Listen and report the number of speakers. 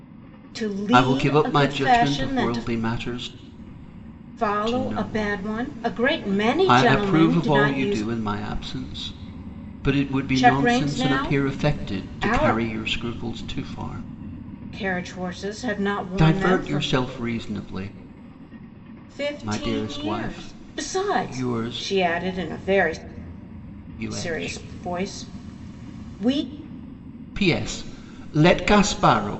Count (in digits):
2